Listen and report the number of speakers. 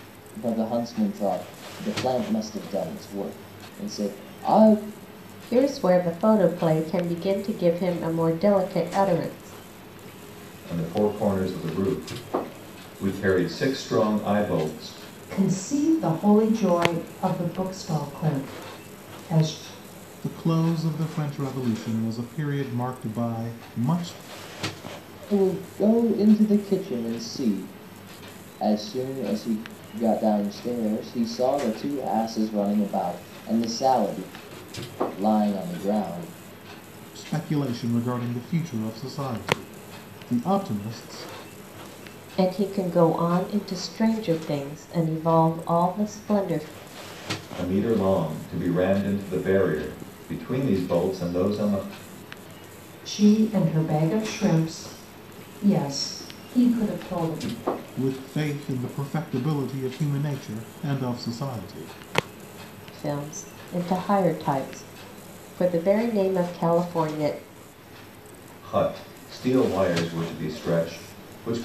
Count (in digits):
5